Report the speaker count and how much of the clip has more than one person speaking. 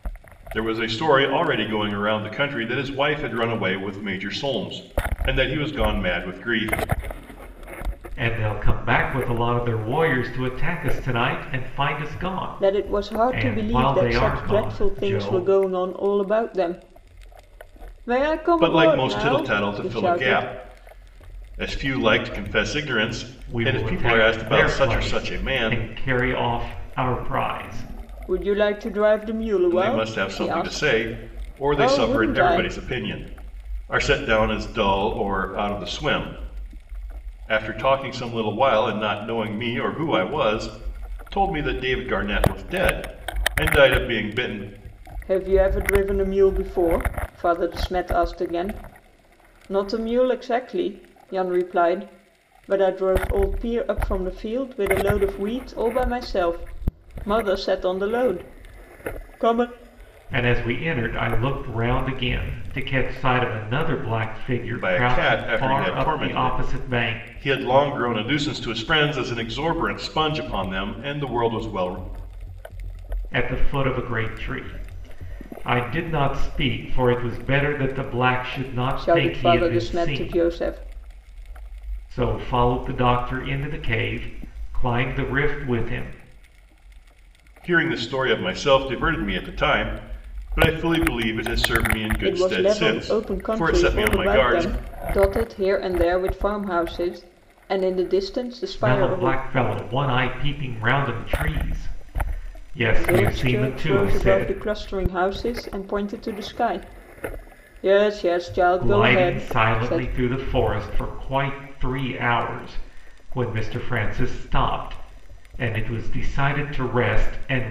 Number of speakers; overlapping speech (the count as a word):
three, about 17%